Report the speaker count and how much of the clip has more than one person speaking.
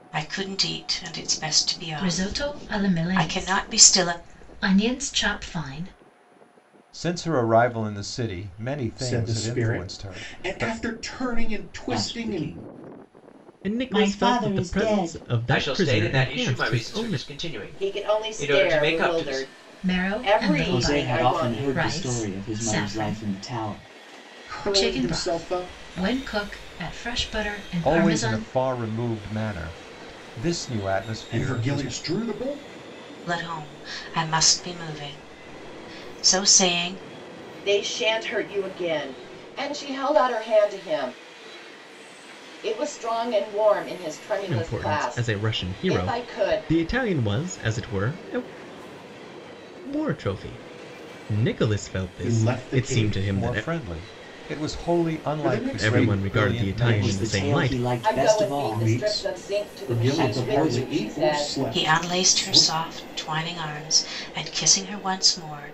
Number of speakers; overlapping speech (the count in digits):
8, about 43%